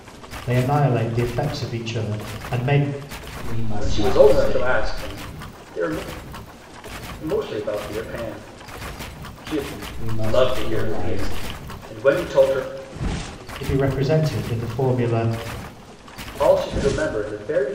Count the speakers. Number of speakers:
three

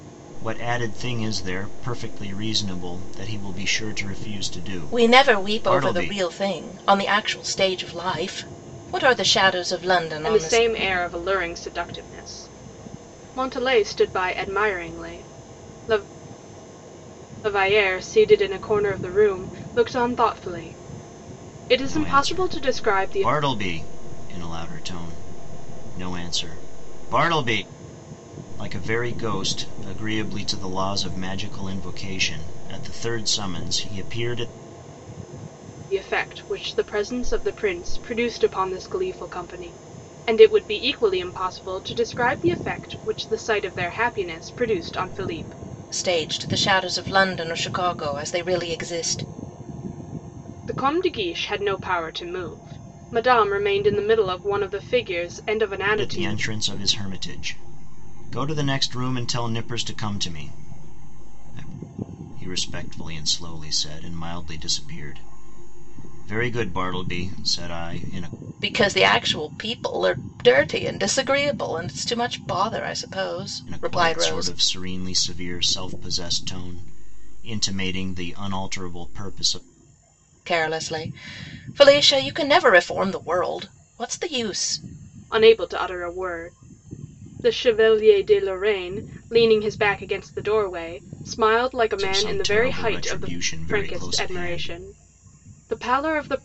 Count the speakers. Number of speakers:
three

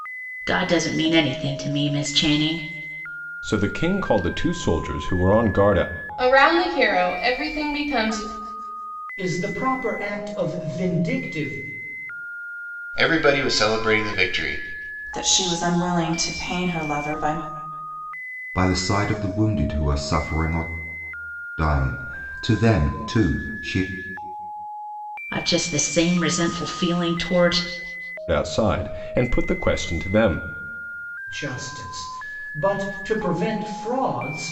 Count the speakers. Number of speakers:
seven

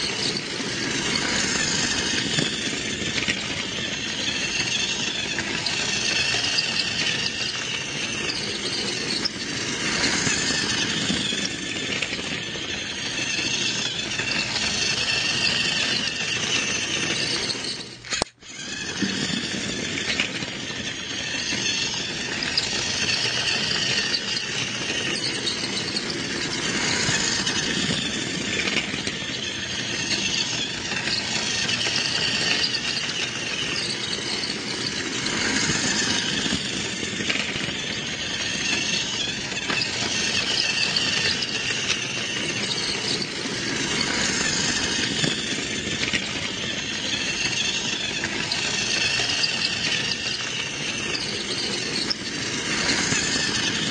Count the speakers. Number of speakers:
zero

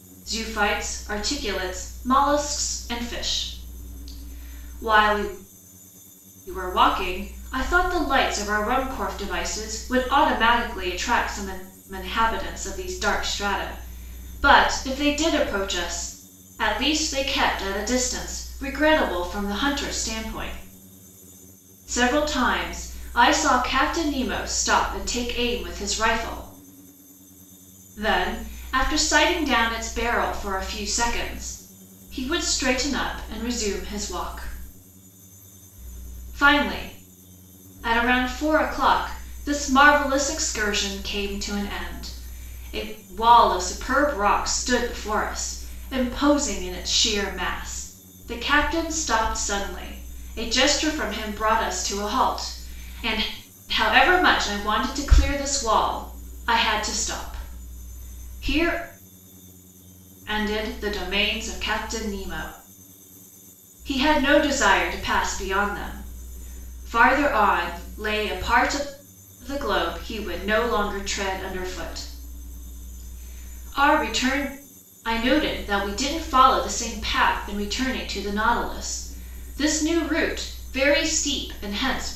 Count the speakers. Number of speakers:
one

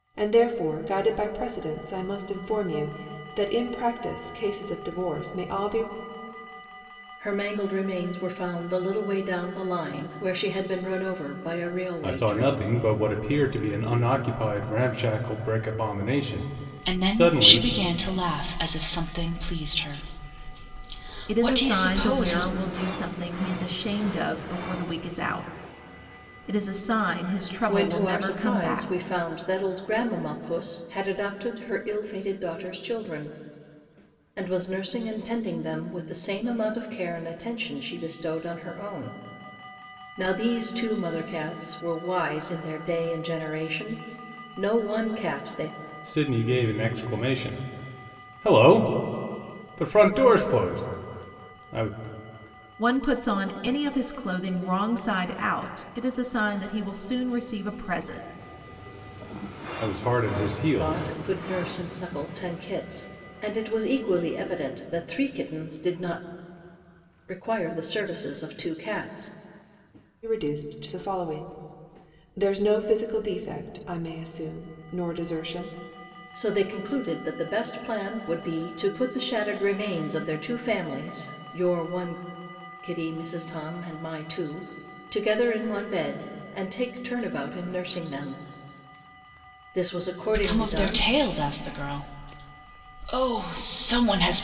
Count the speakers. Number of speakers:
five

